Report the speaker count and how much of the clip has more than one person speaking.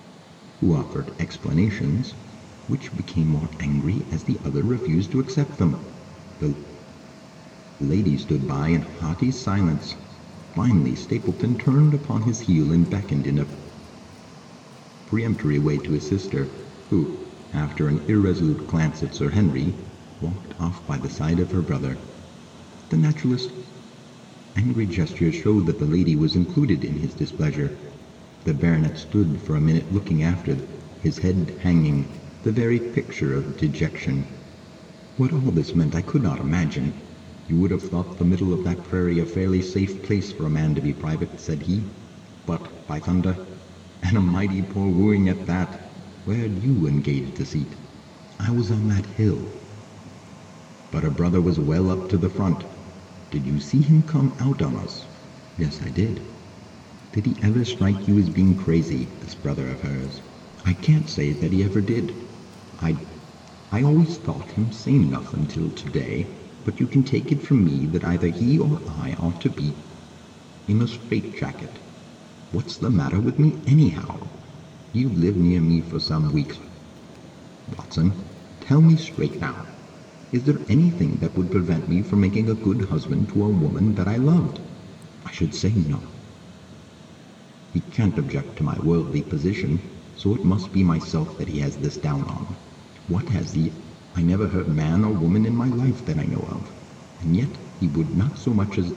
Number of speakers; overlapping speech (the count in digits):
1, no overlap